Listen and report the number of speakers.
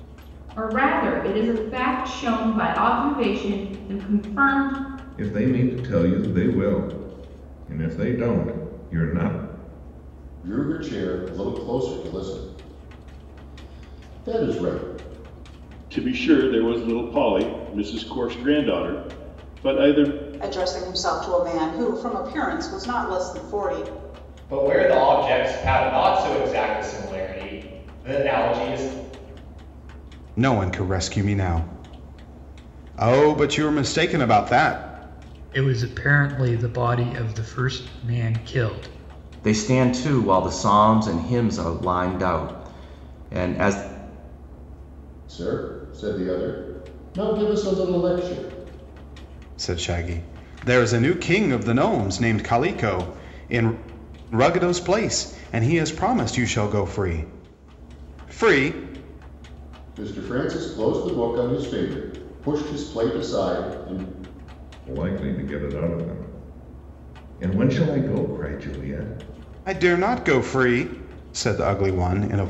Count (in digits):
9